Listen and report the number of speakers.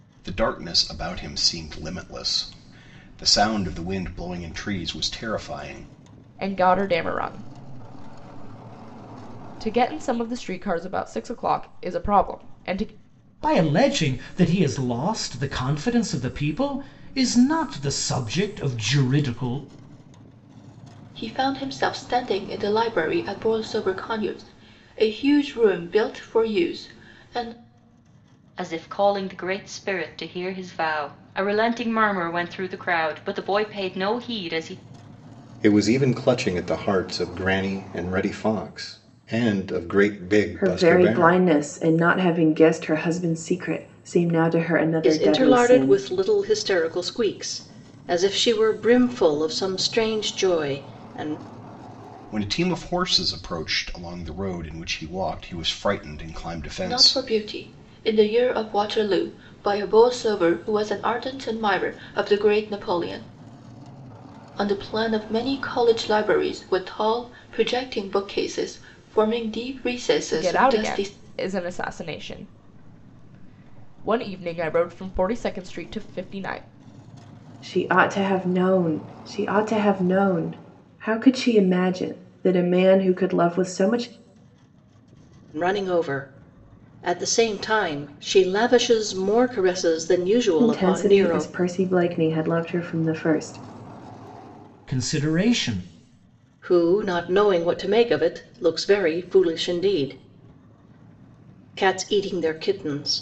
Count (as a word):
eight